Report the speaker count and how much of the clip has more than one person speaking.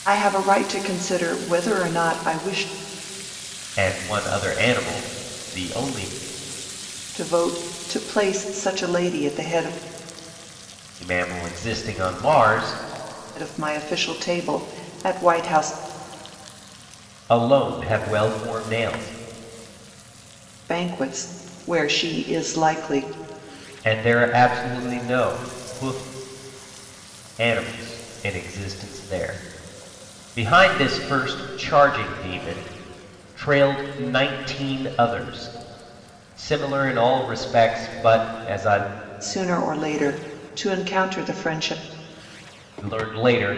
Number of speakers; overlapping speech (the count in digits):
2, no overlap